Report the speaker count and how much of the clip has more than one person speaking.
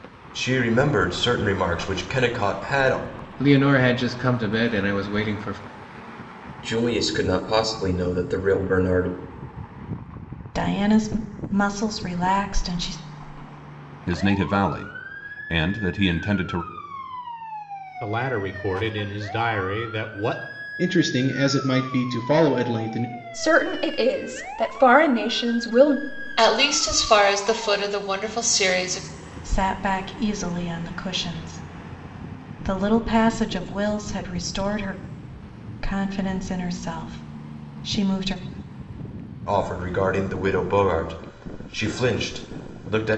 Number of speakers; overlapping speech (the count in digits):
9, no overlap